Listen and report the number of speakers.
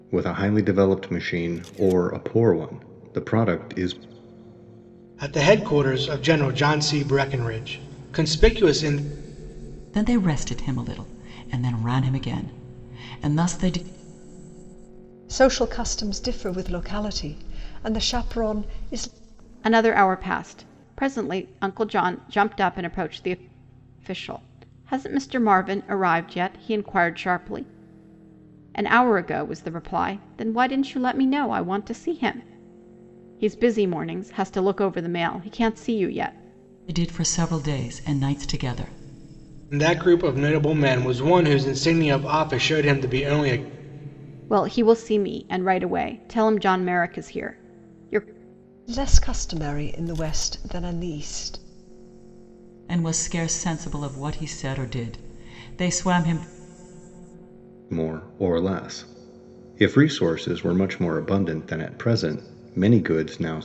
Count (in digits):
5